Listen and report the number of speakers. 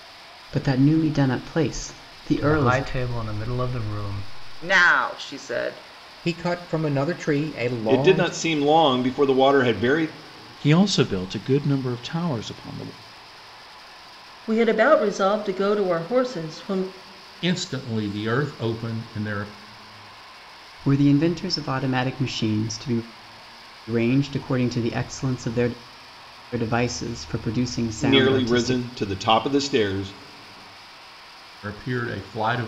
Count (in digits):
8